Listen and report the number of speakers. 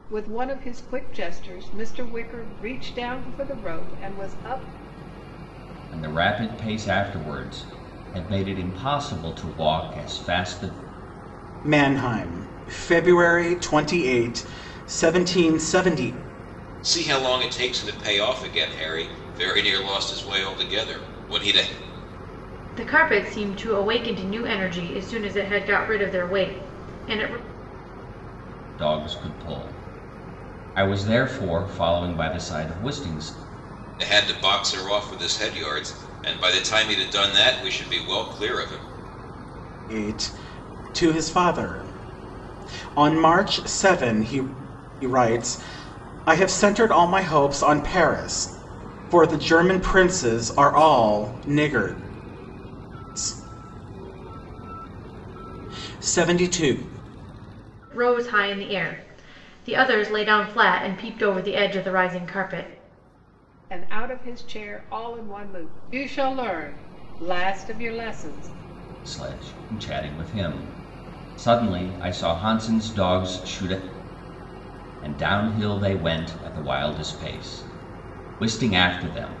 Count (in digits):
5